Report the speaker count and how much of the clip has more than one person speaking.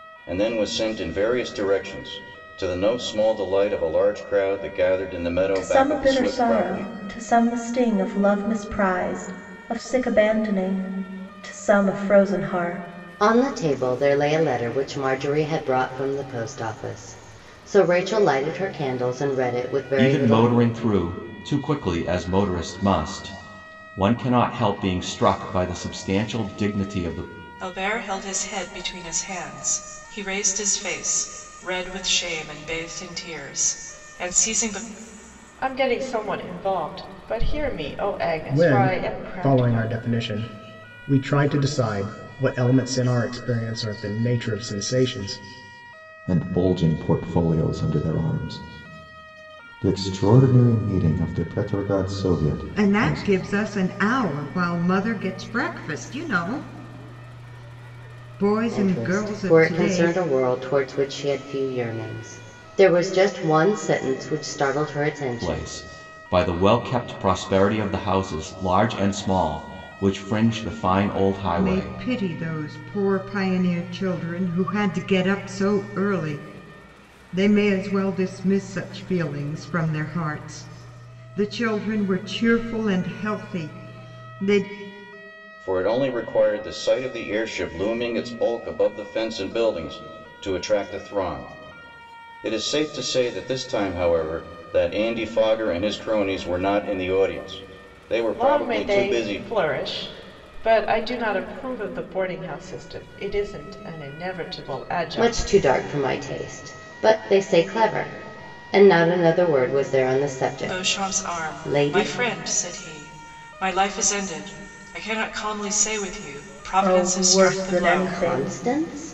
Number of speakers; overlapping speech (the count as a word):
nine, about 9%